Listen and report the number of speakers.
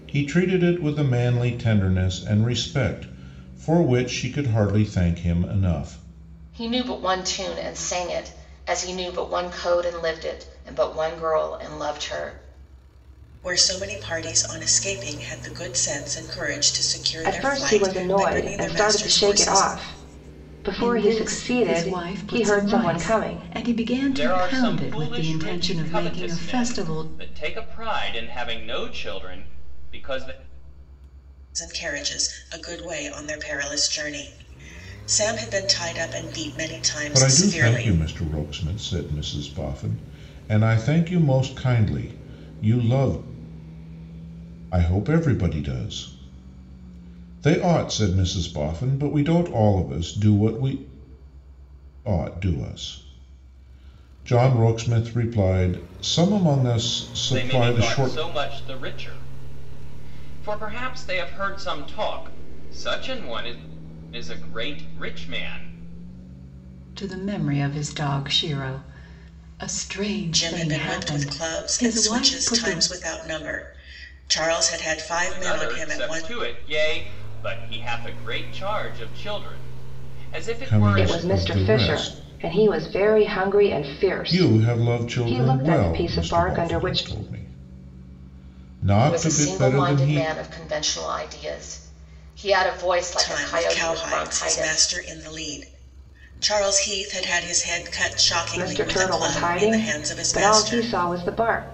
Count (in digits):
6